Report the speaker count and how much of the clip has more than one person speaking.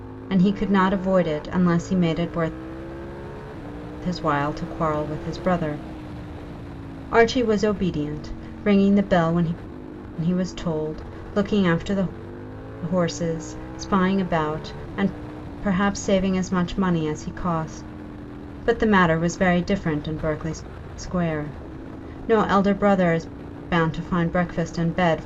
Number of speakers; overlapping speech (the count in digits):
1, no overlap